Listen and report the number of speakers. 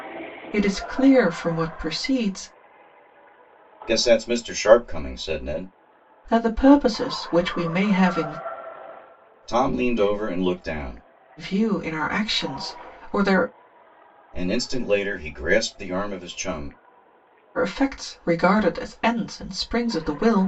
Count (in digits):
2